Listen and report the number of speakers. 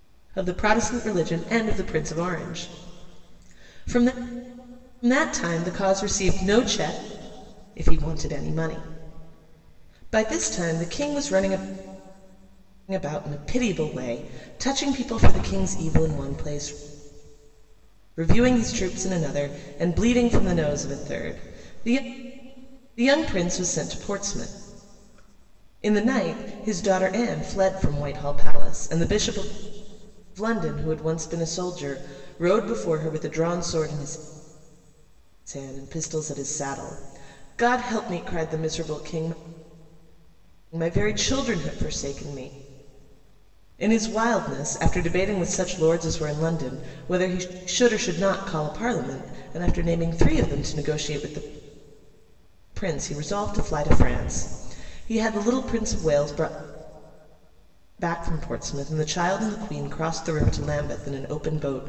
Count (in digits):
1